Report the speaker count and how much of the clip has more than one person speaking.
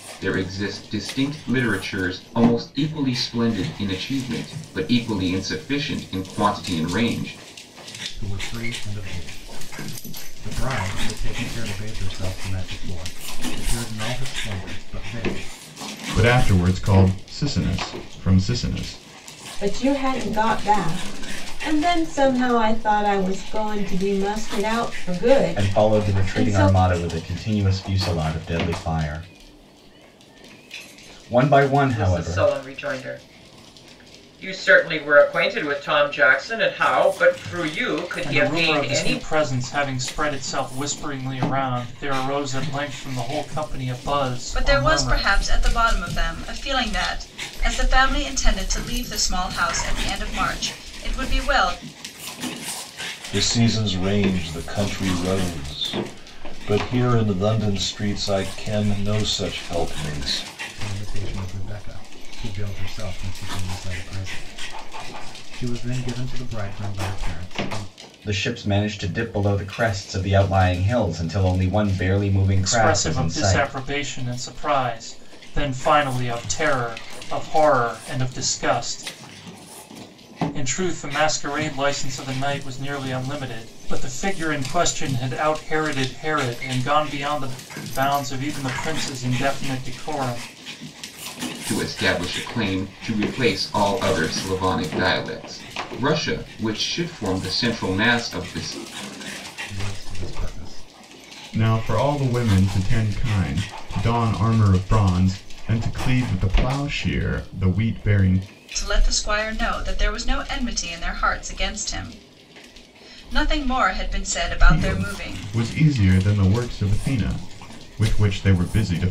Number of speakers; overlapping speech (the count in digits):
9, about 5%